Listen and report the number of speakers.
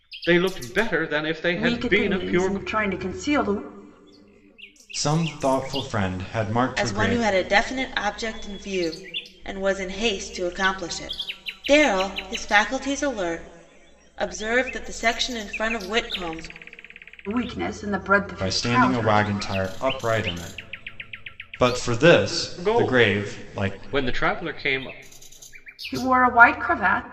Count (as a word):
four